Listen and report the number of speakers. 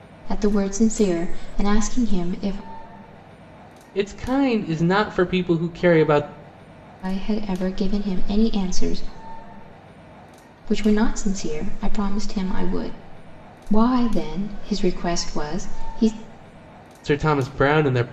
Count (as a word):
two